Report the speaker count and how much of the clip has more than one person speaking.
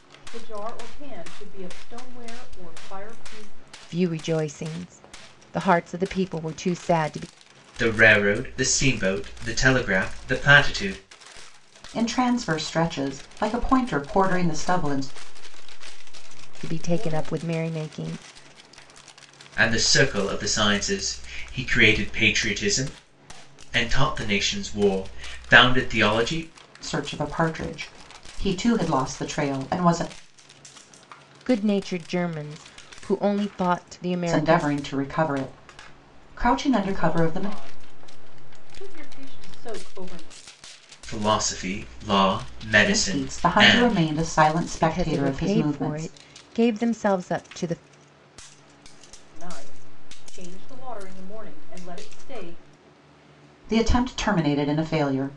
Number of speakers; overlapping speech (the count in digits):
4, about 10%